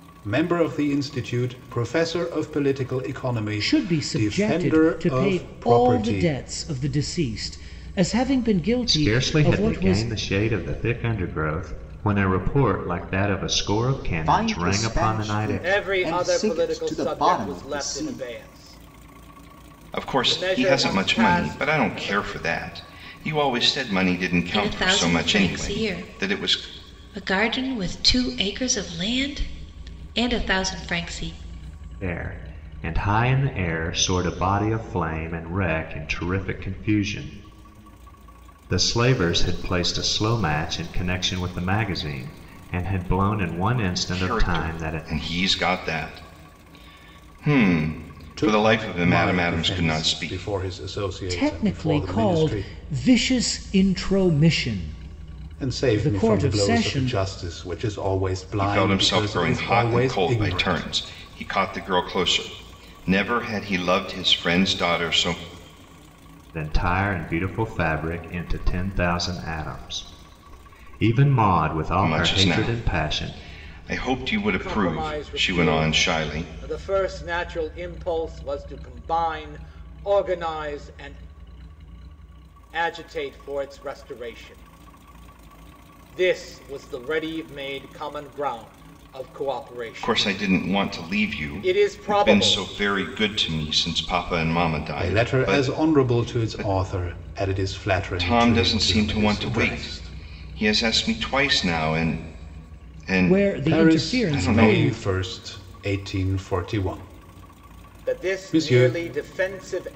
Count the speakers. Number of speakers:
7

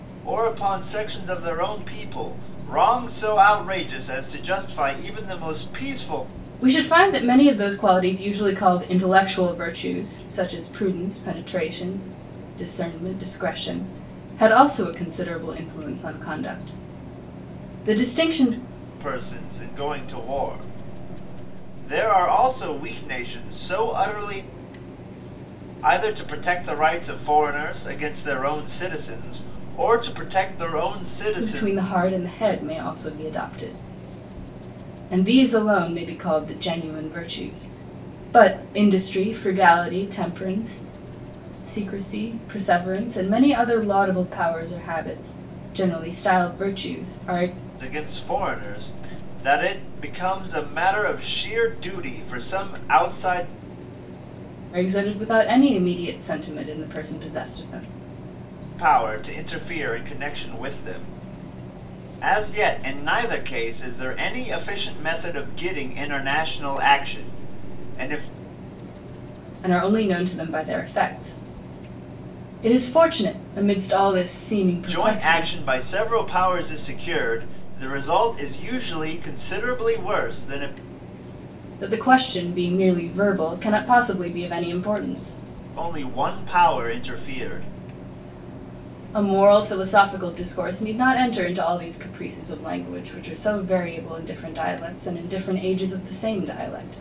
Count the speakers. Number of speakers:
2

